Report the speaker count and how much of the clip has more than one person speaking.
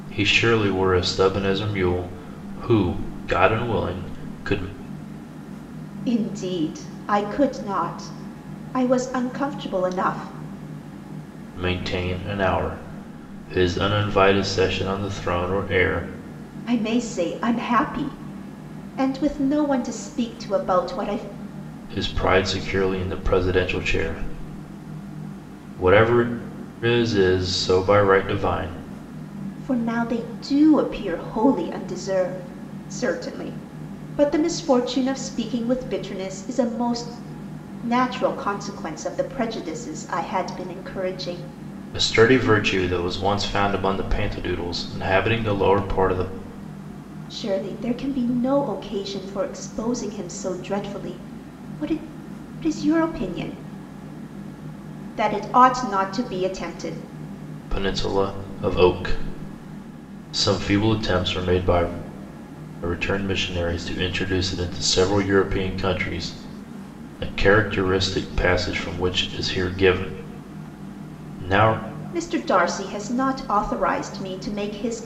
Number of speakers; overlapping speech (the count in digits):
2, no overlap